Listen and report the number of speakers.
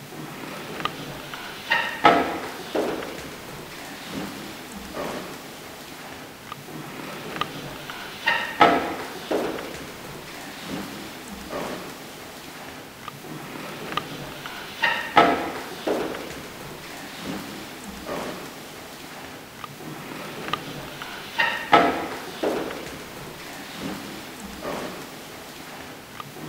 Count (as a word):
zero